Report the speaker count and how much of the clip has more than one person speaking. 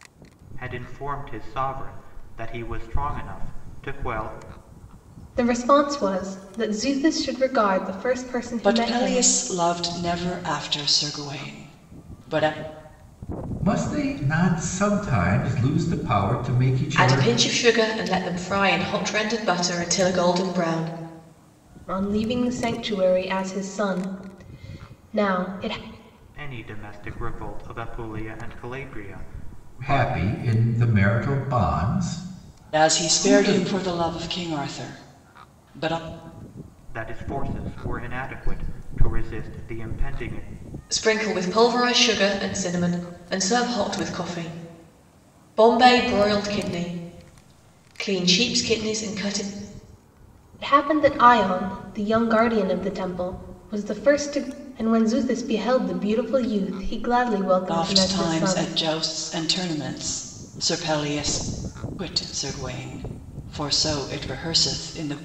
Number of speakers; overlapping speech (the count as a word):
five, about 5%